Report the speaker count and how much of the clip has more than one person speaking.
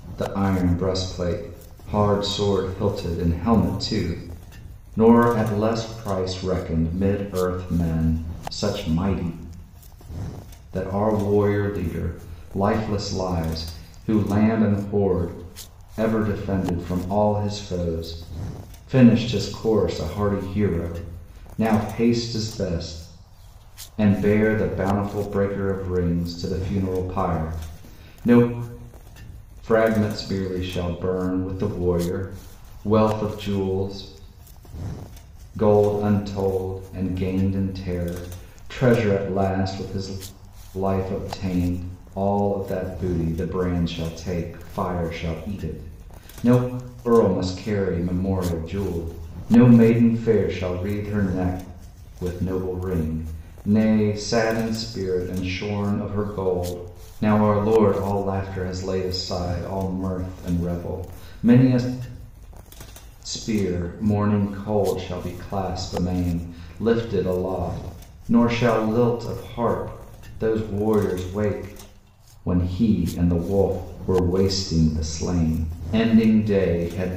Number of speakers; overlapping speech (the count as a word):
one, no overlap